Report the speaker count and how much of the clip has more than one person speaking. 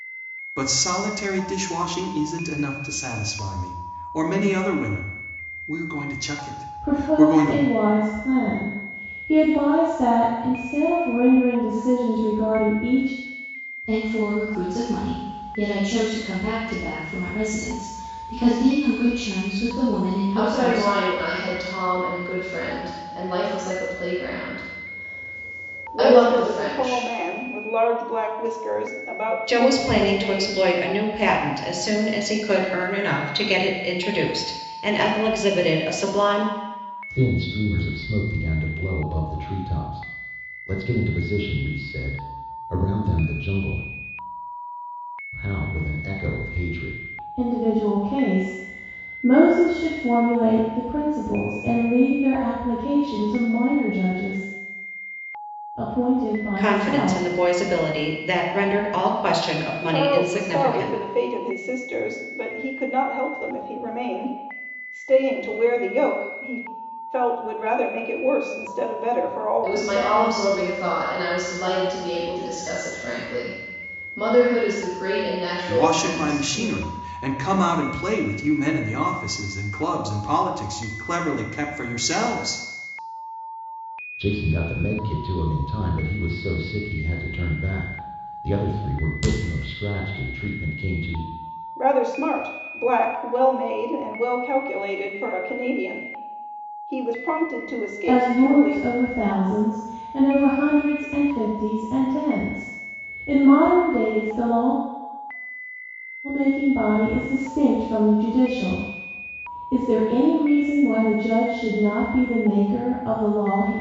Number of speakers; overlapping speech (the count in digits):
7, about 8%